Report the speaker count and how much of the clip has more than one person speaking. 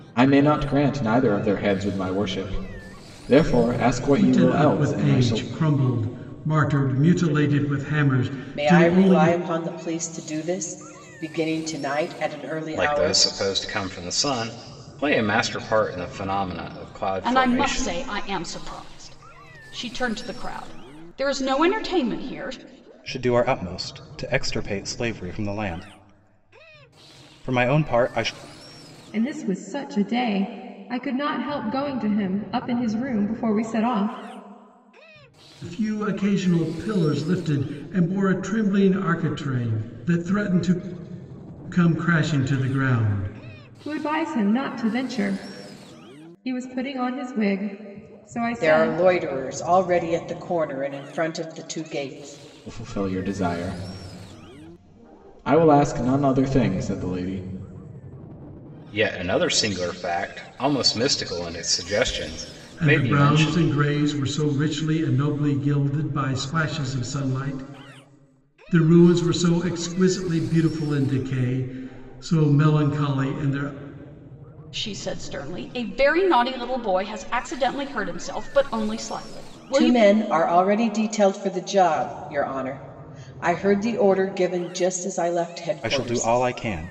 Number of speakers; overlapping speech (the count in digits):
7, about 7%